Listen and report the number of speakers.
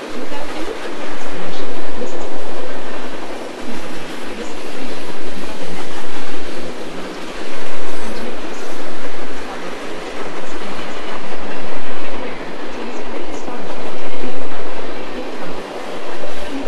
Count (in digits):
1